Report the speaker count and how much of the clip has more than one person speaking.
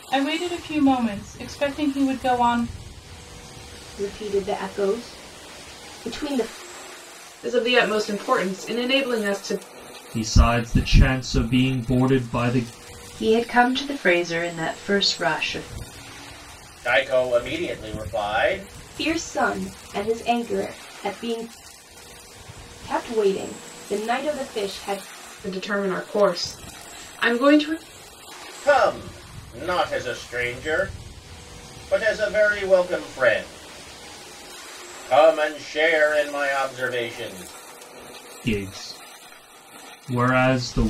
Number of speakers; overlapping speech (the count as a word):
six, no overlap